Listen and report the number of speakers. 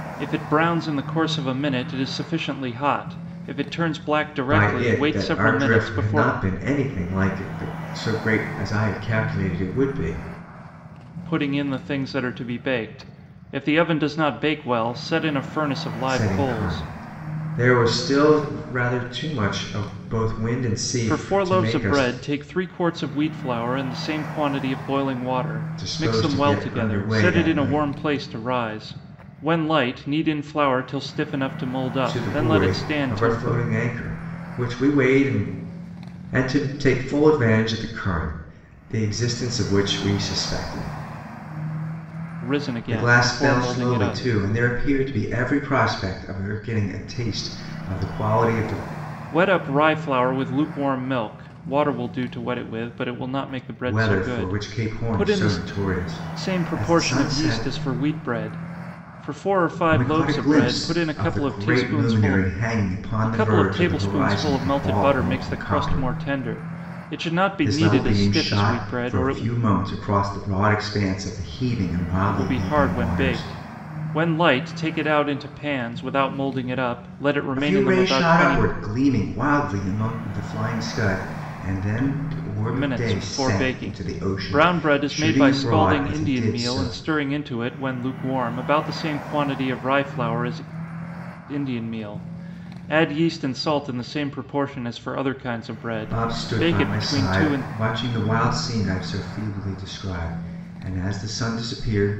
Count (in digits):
2